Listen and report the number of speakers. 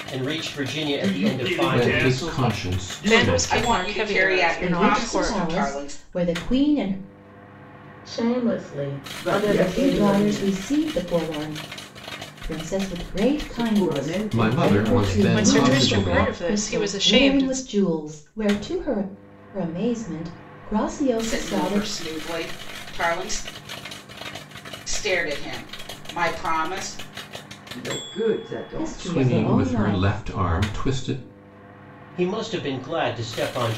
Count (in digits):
8